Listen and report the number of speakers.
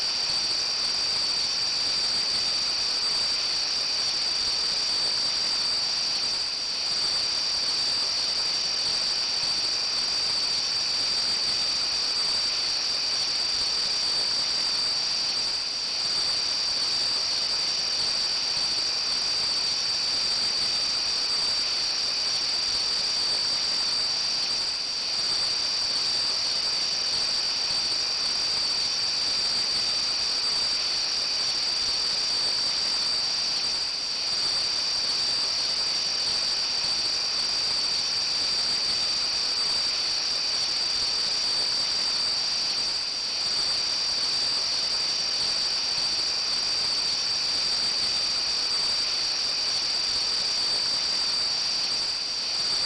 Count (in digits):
0